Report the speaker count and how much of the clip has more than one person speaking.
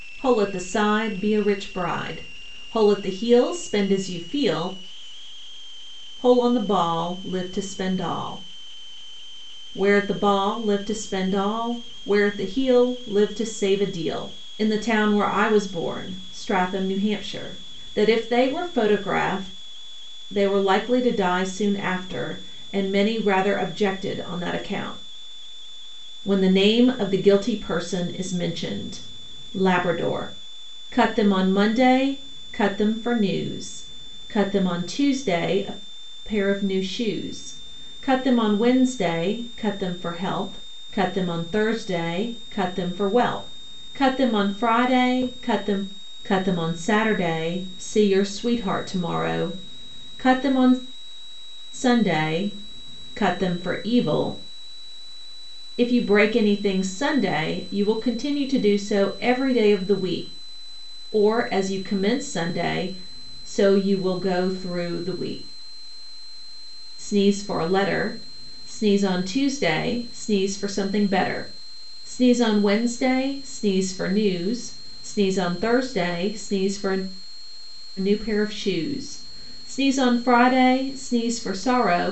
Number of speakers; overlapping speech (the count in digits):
1, no overlap